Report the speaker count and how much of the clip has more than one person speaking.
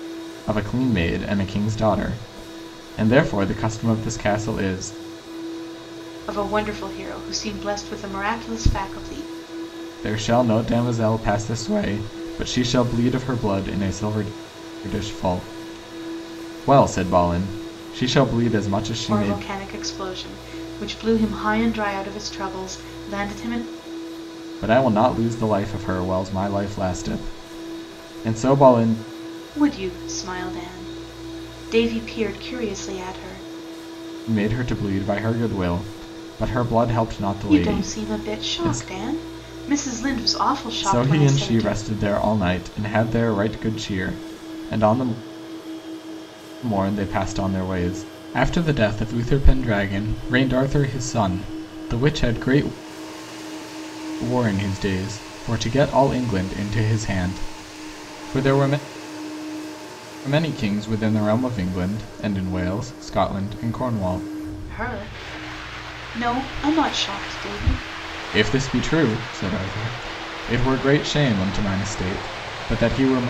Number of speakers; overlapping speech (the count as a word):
two, about 4%